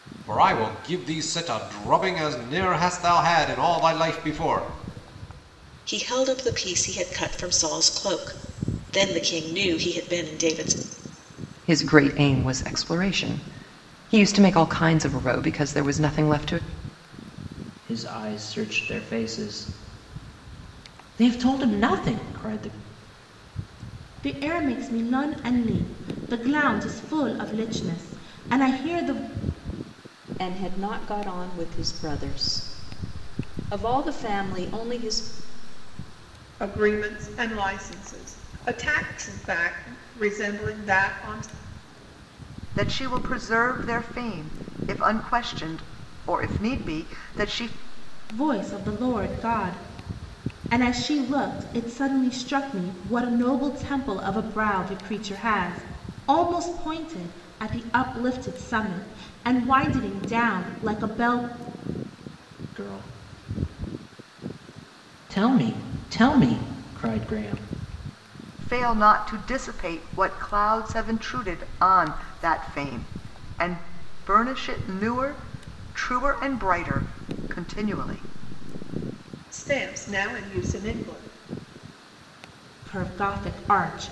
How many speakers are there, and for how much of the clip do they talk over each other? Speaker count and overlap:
eight, no overlap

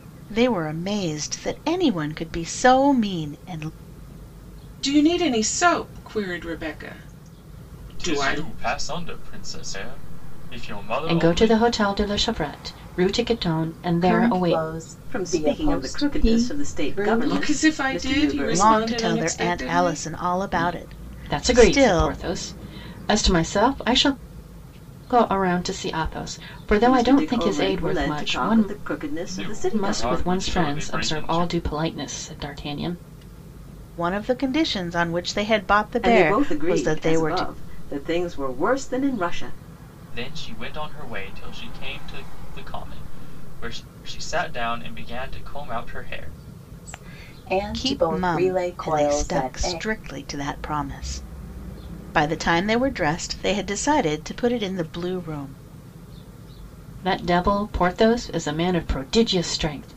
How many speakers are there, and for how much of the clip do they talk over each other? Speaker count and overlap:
six, about 27%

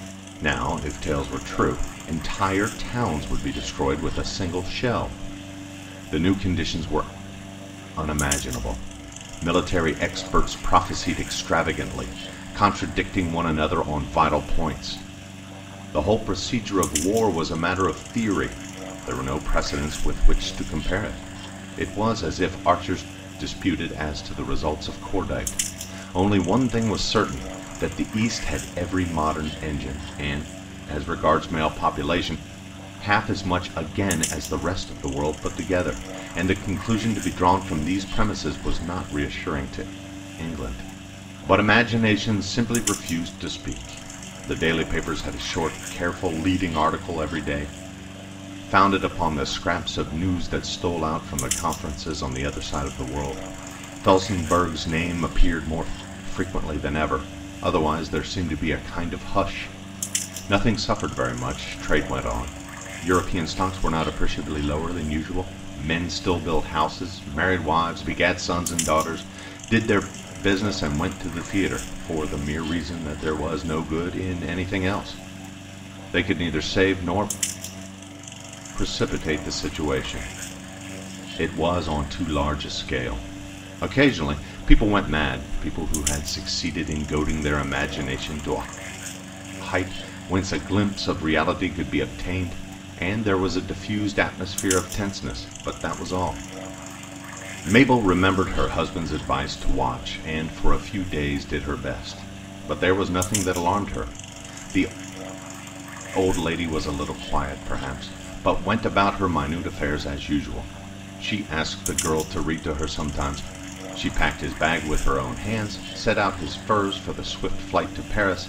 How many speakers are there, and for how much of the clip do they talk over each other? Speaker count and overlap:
one, no overlap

